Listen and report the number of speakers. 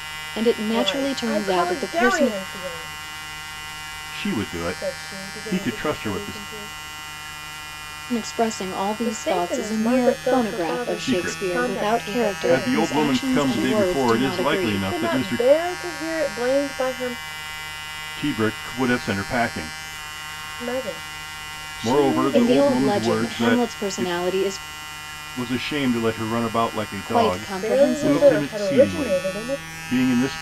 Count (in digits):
3